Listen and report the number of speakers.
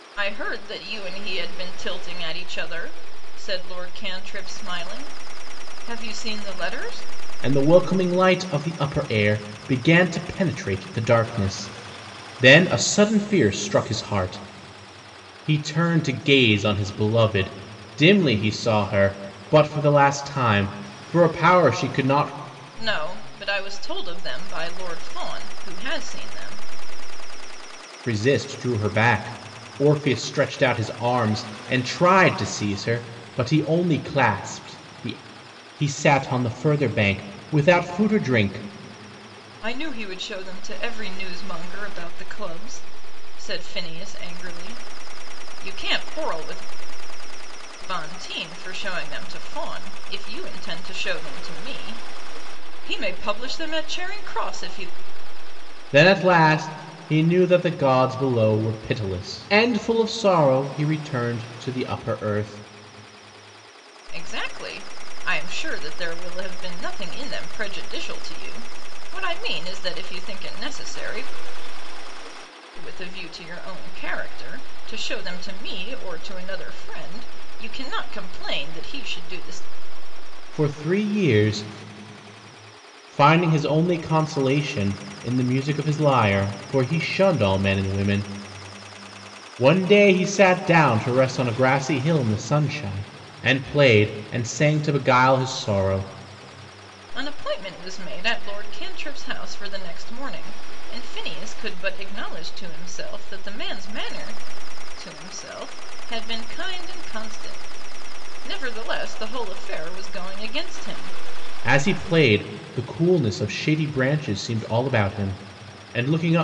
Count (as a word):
two